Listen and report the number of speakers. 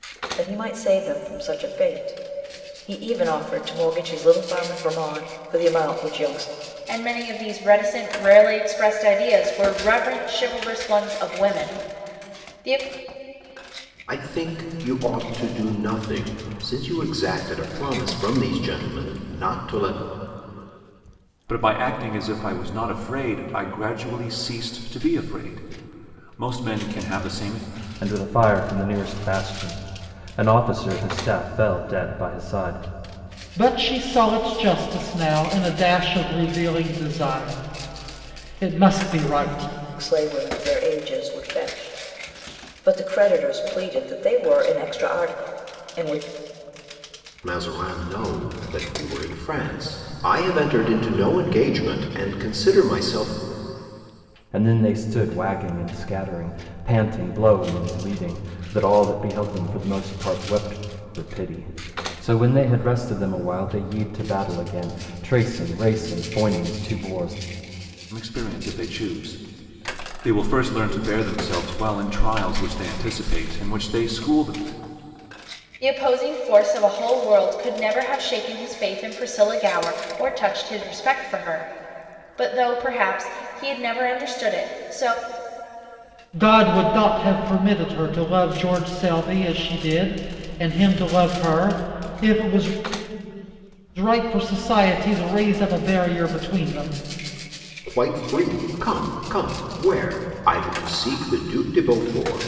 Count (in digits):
6